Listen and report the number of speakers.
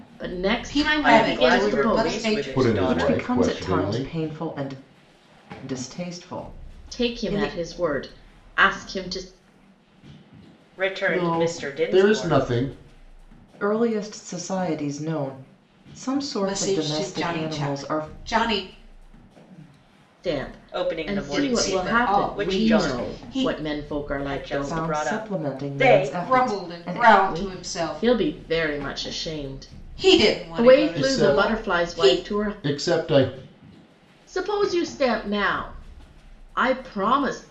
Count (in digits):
5